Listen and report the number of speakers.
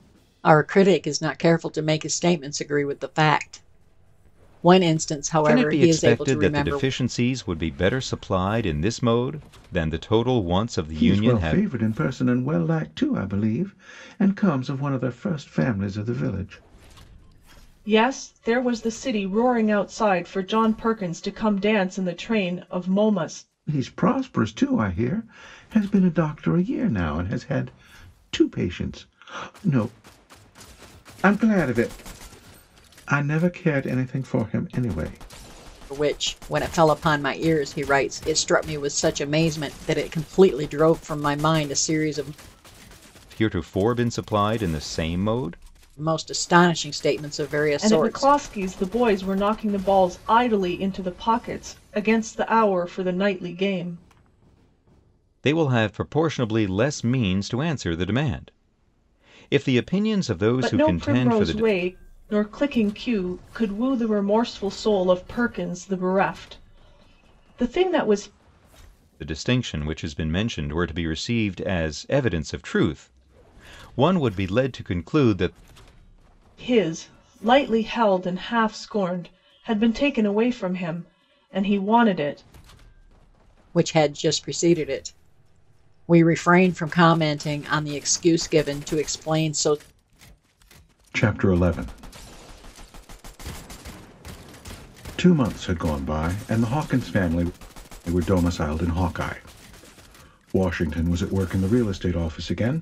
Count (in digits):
4